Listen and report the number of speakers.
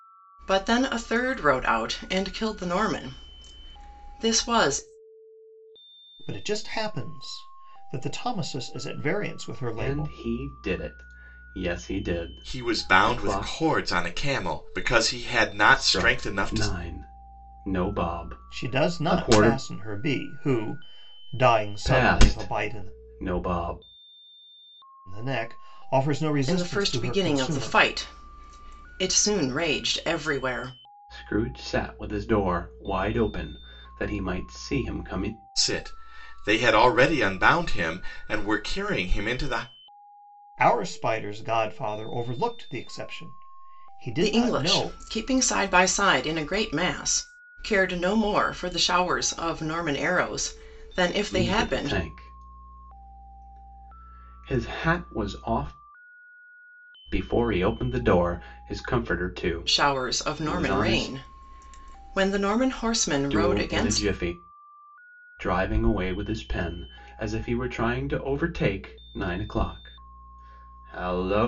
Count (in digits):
4